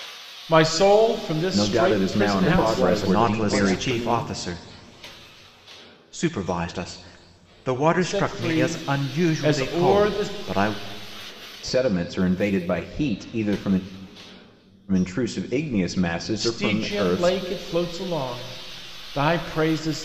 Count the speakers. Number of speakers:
4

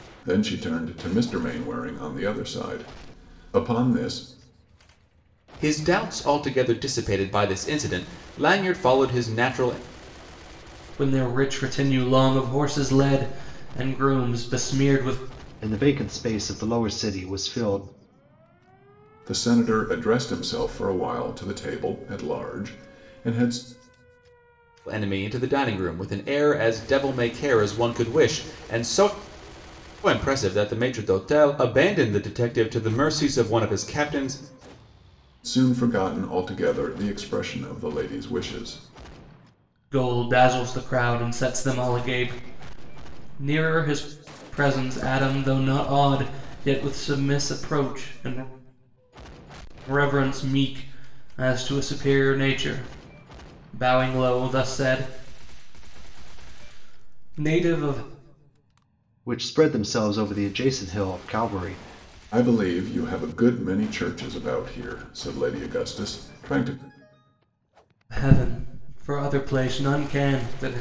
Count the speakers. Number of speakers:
4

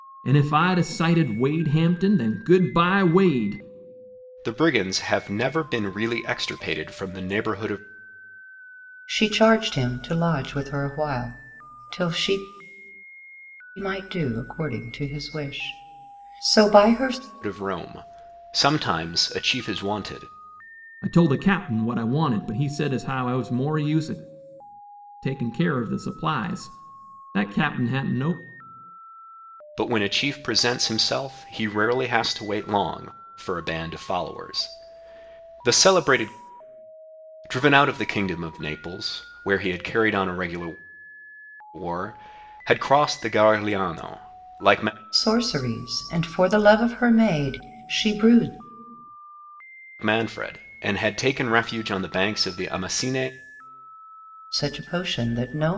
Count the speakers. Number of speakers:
3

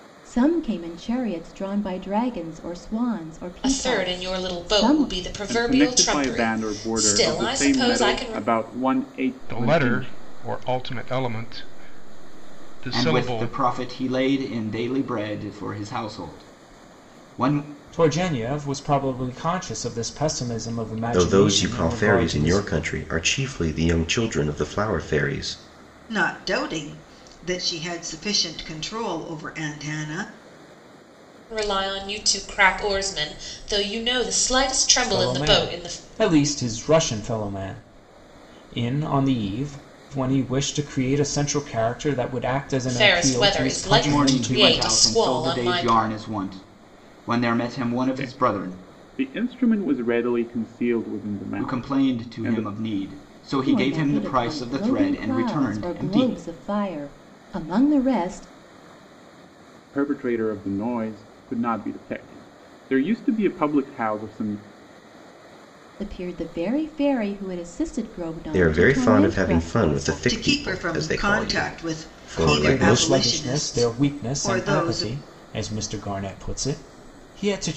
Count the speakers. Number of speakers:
8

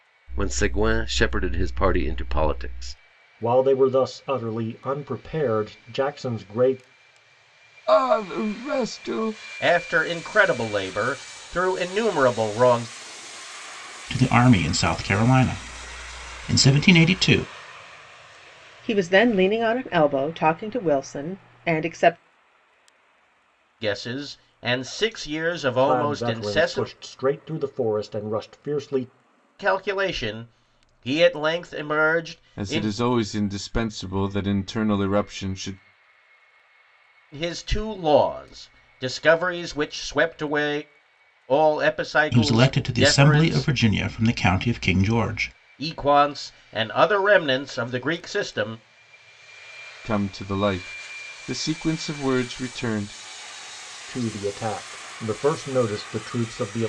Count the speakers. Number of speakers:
6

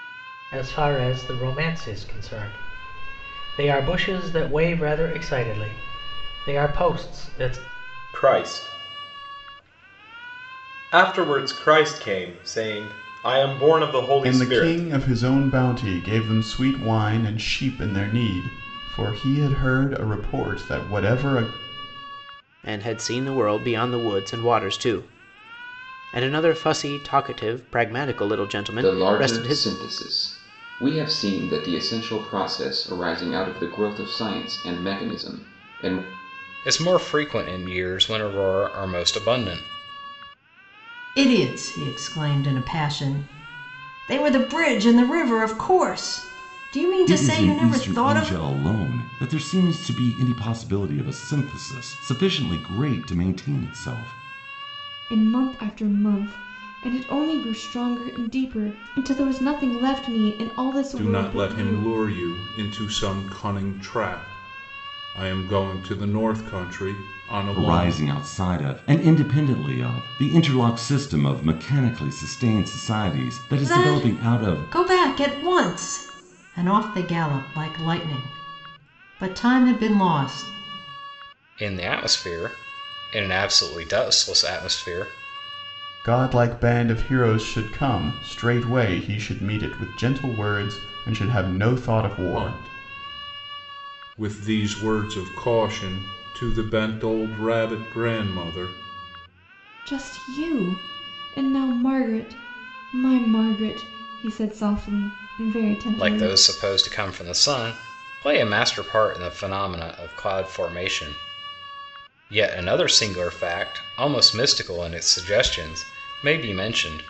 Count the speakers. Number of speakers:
10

